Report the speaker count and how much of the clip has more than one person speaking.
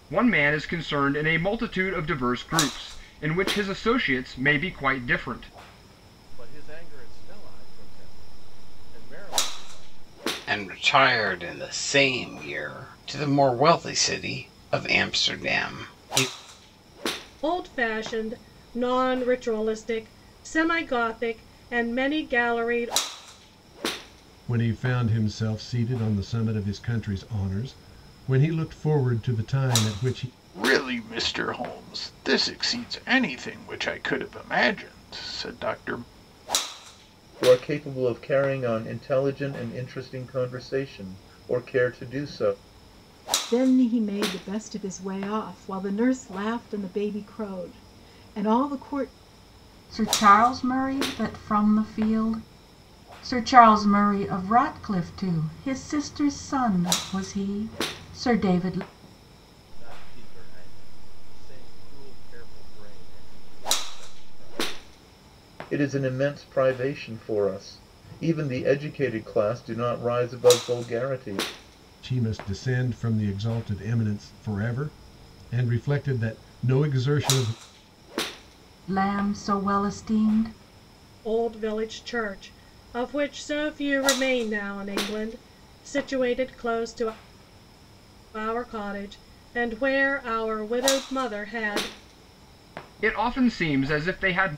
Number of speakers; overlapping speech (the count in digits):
9, no overlap